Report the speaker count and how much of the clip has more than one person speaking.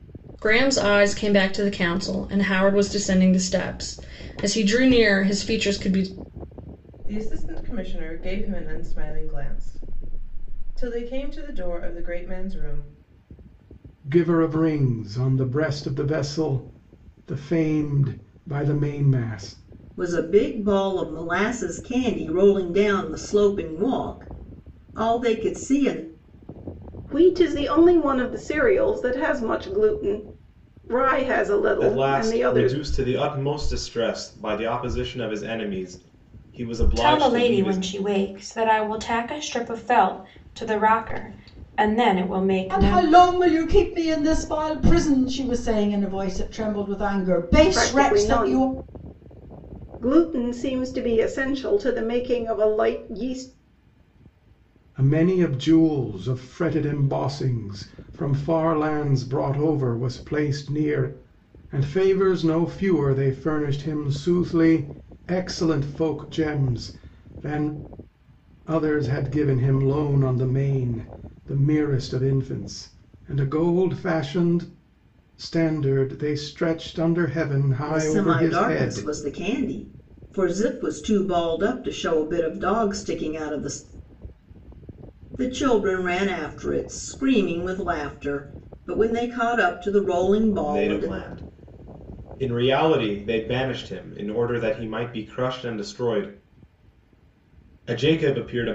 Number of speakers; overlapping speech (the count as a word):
eight, about 5%